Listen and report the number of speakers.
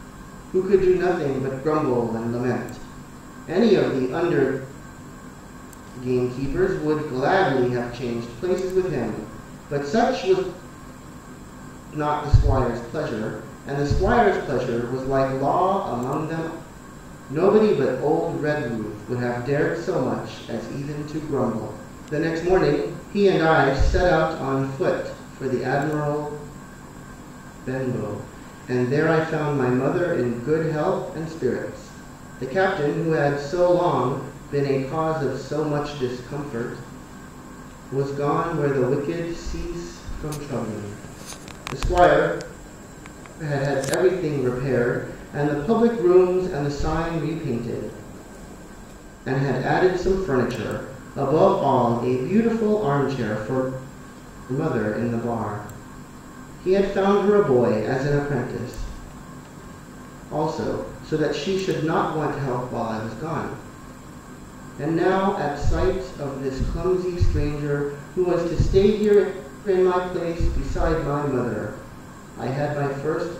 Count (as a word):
one